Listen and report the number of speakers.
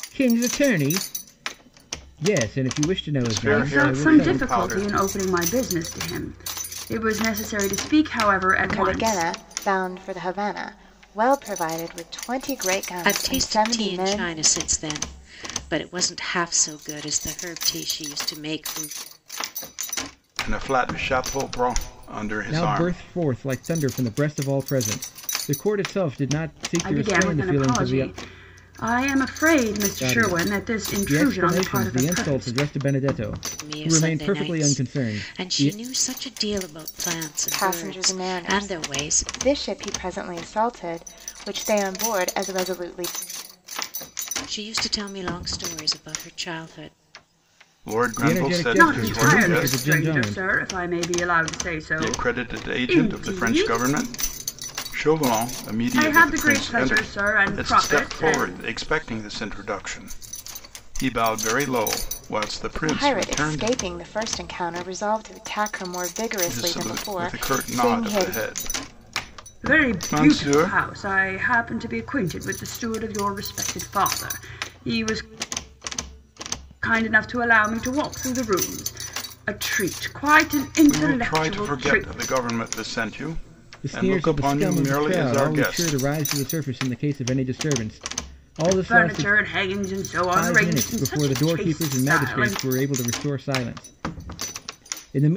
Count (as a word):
five